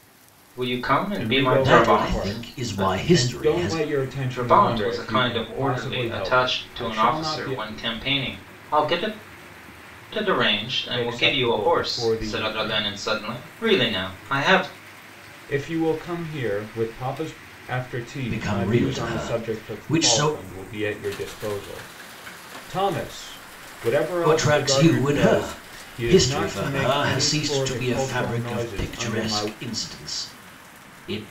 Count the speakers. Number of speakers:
3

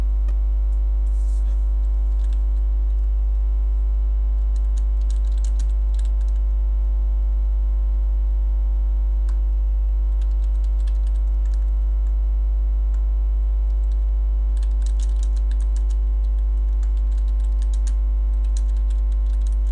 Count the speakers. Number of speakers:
0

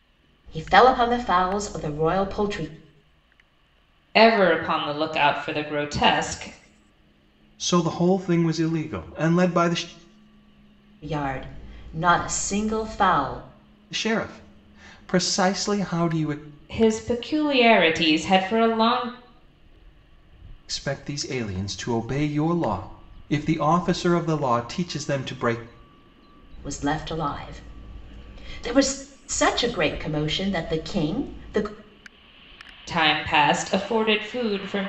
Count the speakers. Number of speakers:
3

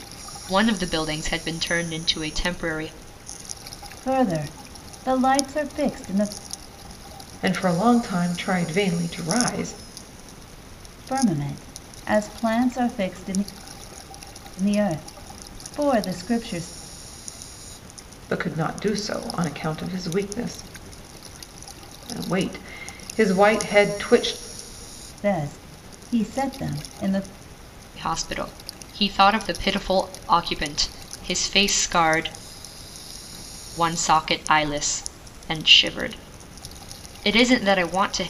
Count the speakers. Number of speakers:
3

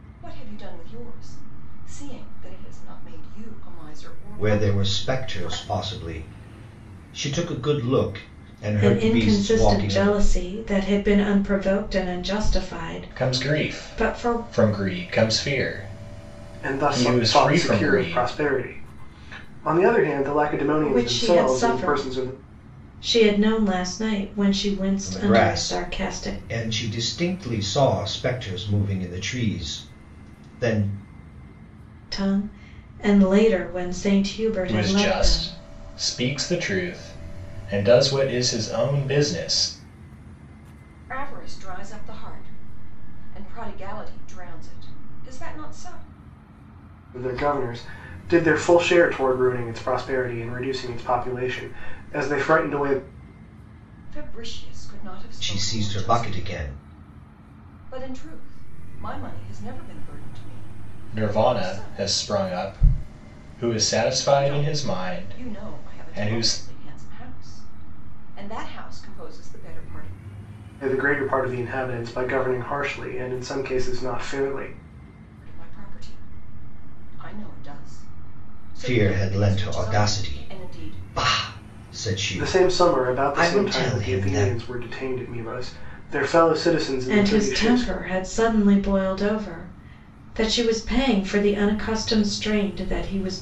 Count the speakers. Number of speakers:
5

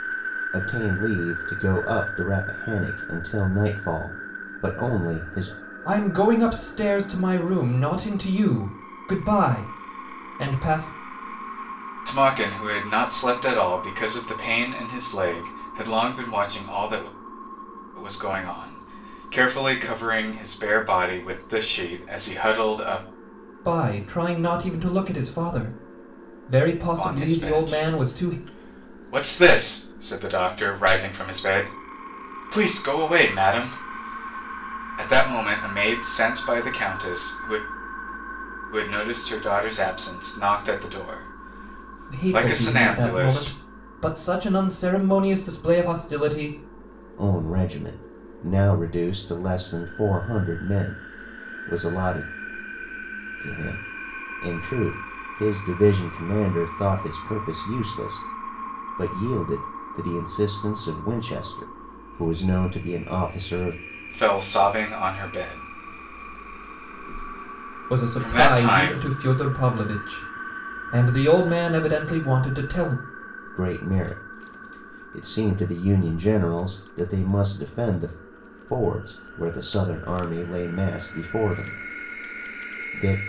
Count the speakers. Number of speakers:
3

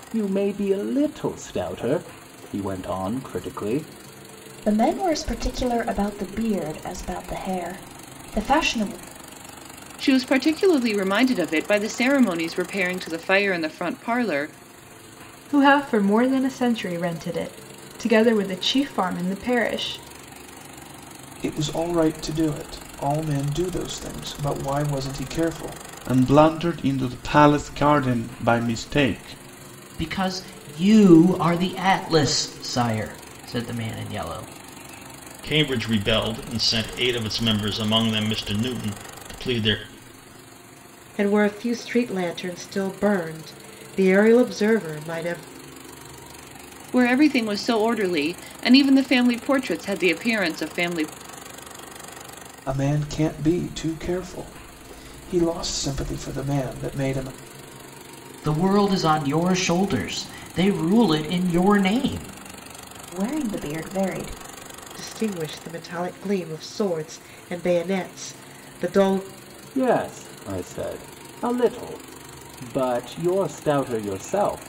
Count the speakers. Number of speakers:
9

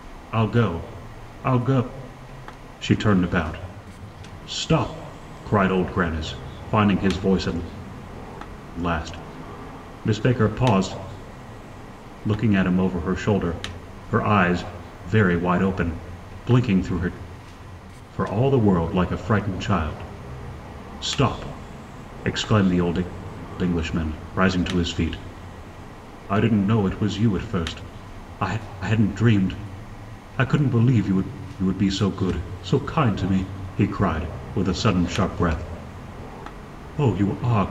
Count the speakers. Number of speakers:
1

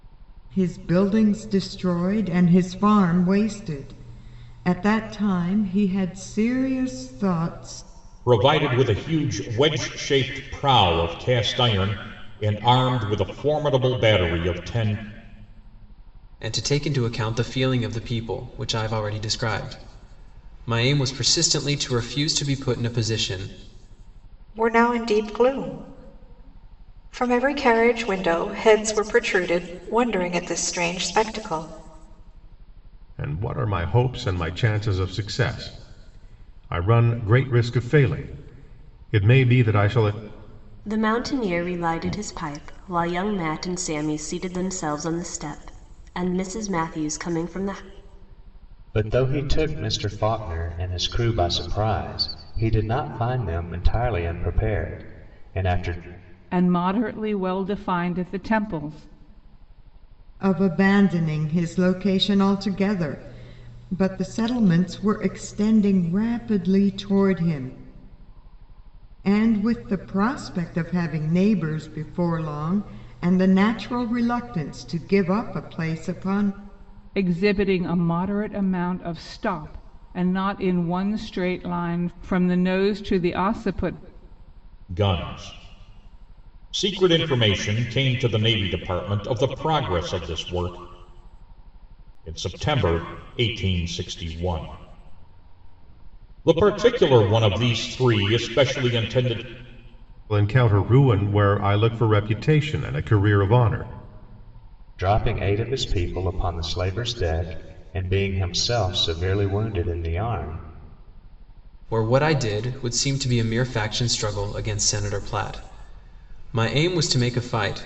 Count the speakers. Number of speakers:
8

